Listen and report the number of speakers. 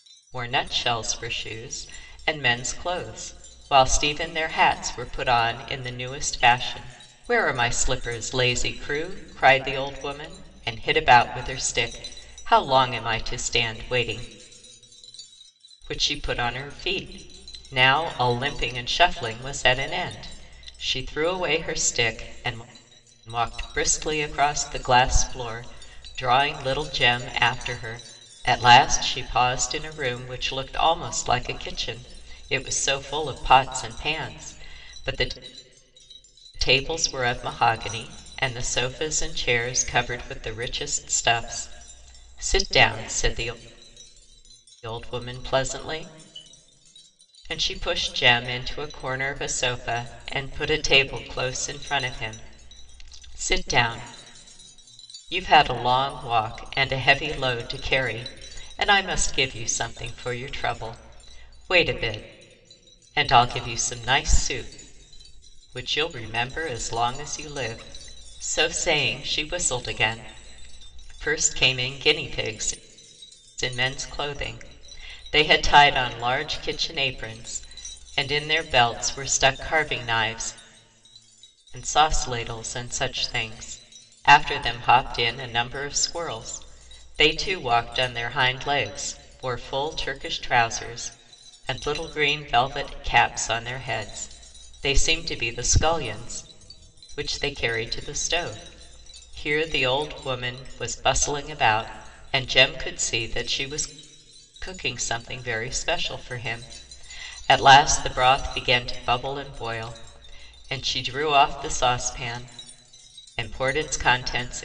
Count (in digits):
1